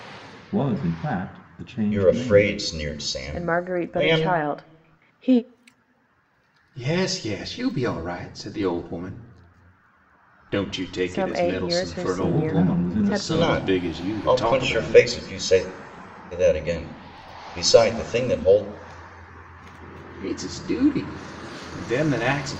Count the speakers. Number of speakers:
four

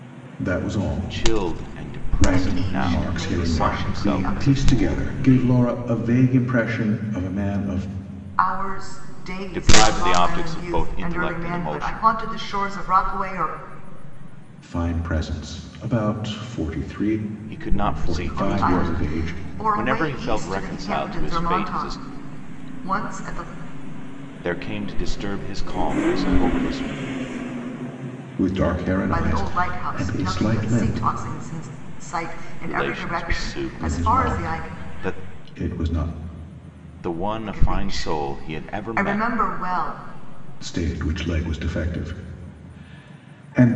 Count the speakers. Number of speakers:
three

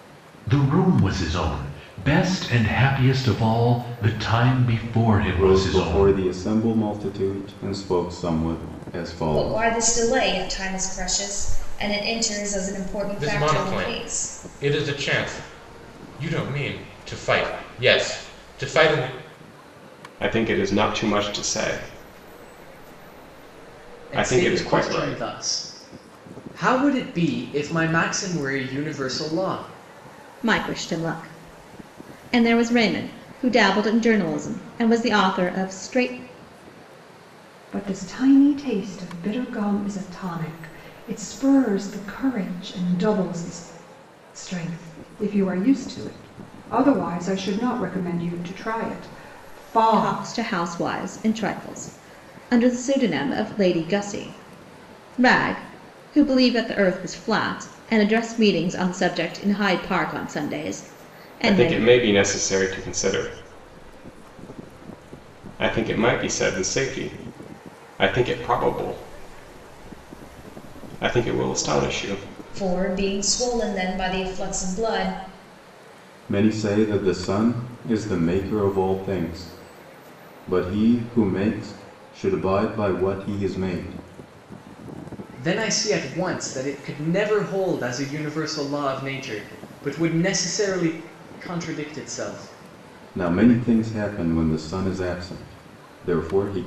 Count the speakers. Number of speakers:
eight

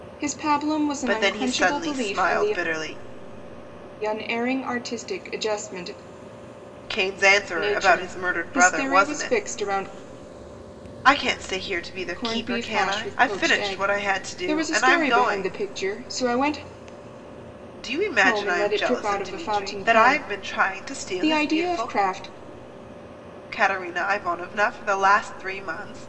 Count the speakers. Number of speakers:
two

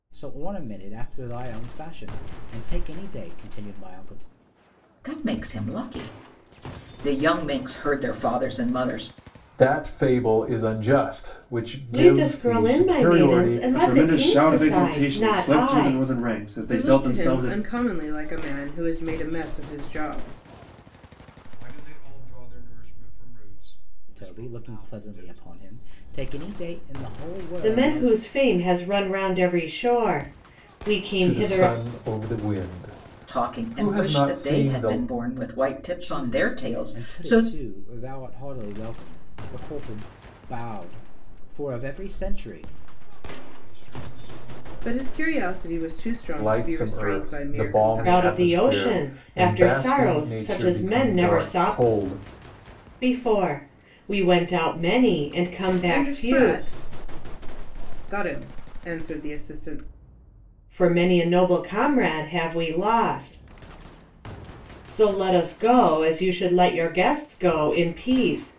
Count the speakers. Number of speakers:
seven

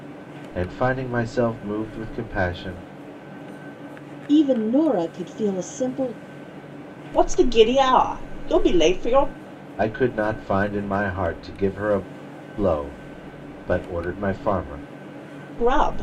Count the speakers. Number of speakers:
three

